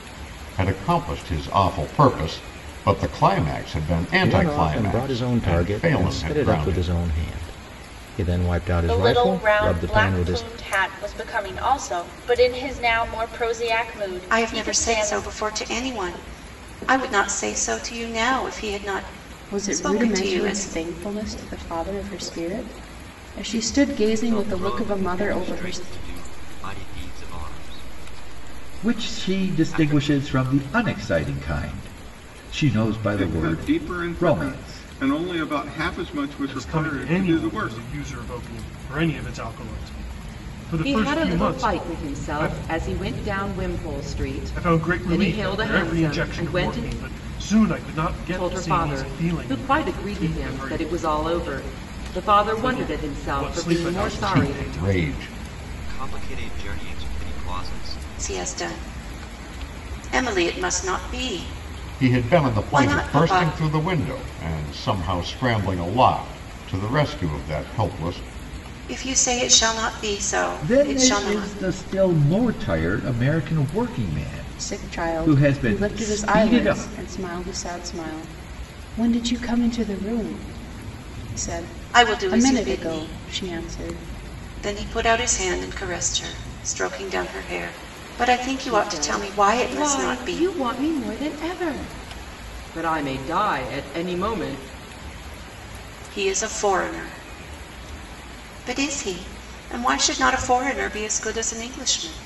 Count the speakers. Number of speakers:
ten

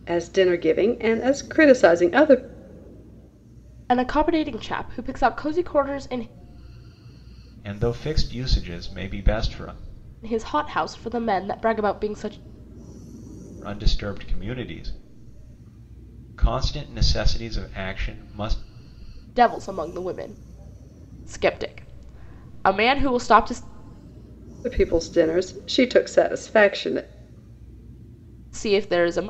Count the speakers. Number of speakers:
three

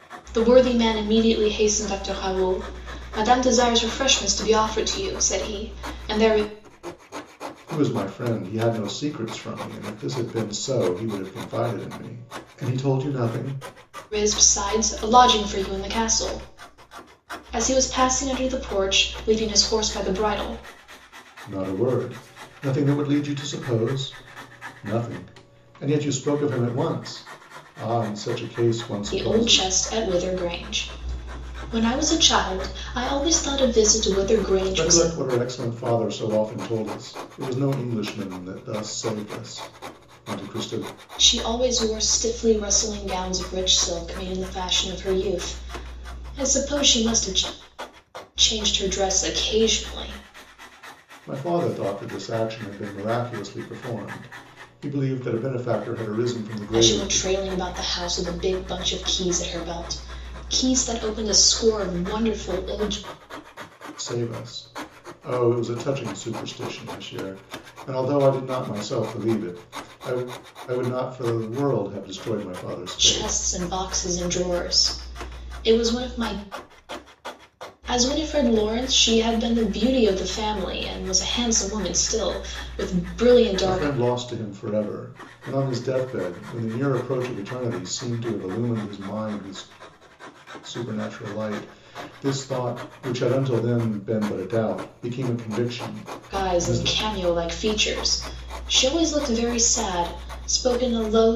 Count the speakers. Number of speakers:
two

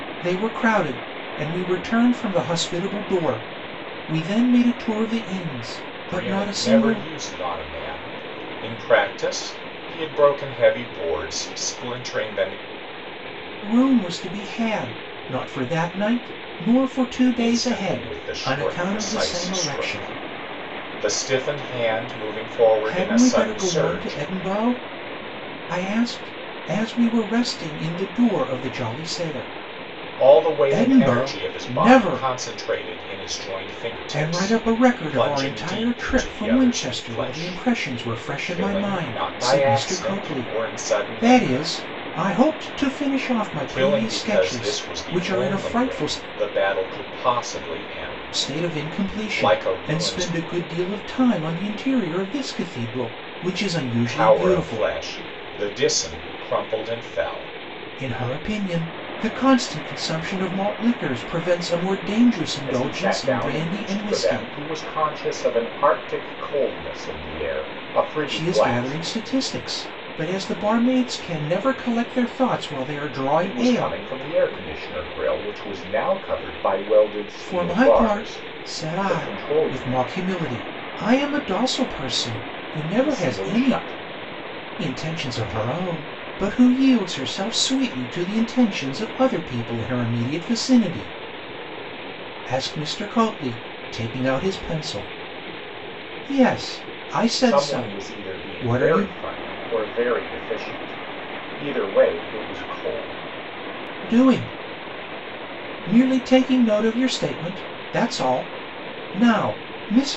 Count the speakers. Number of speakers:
two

